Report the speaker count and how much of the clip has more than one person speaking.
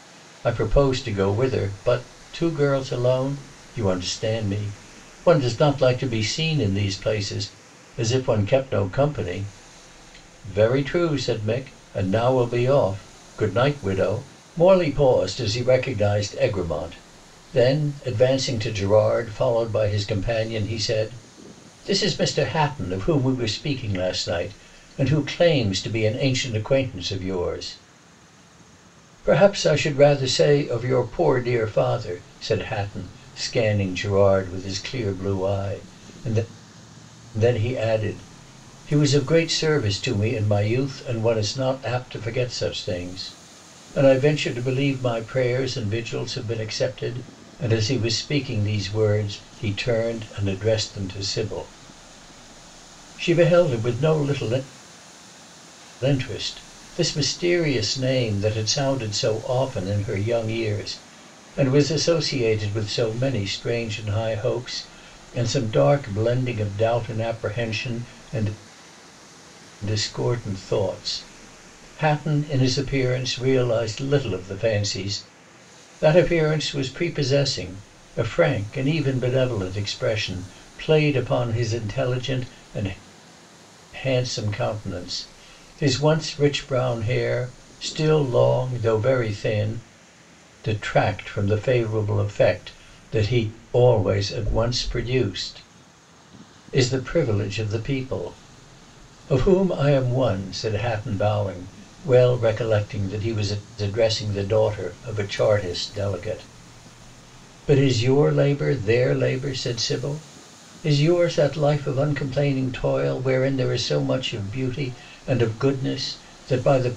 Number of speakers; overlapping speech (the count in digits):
1, no overlap